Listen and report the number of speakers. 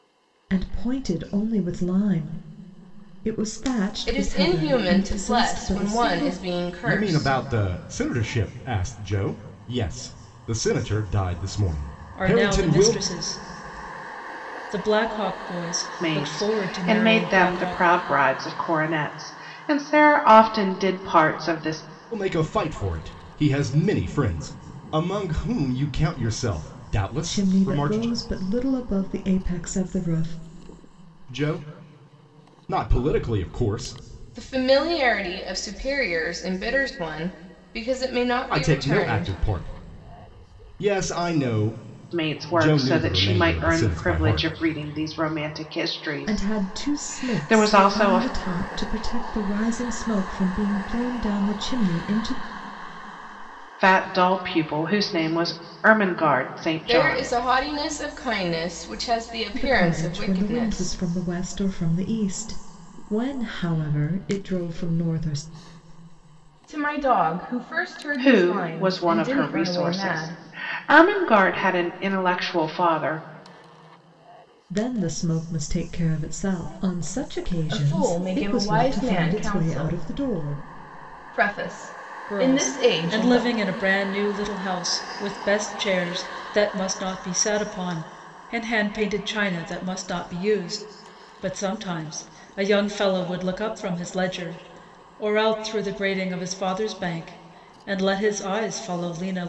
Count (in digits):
5